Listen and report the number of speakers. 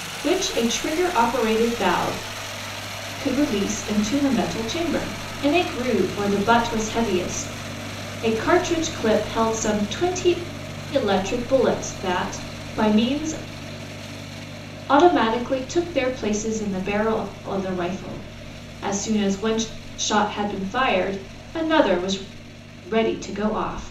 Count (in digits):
1